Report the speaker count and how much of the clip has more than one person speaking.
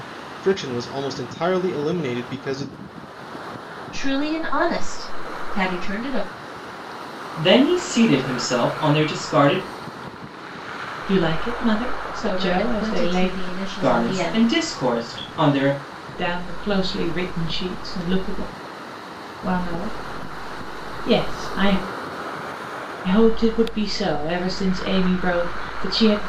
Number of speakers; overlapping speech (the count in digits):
4, about 8%